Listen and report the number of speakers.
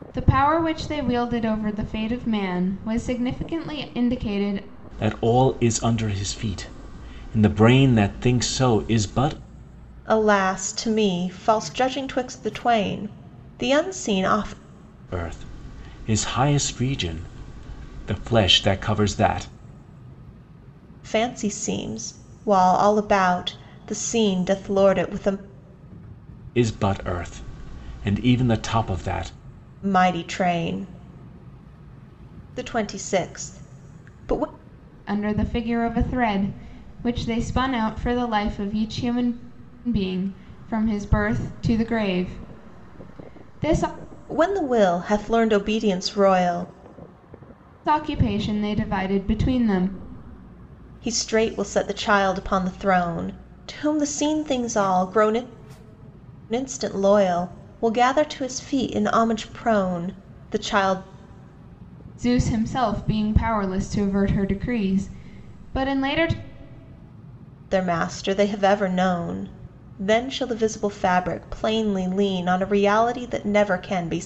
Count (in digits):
3